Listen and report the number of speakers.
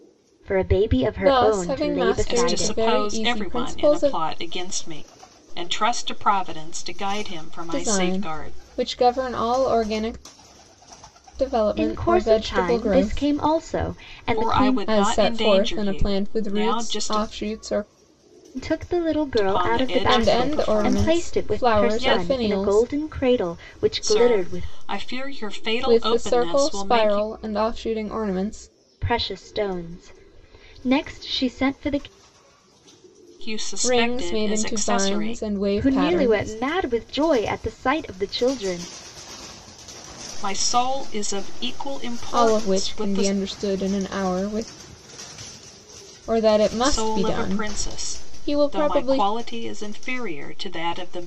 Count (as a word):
three